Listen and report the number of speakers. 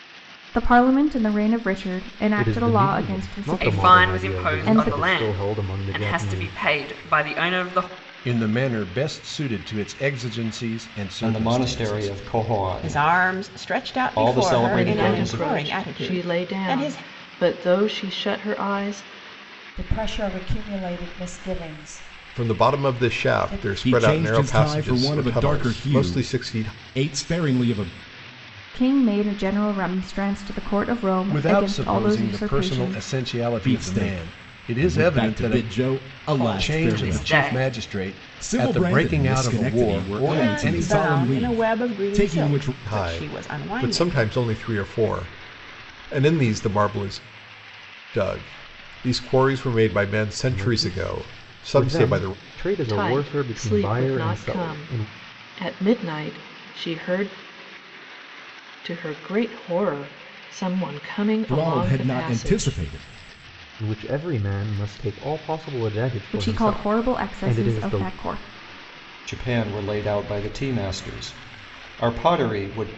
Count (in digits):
10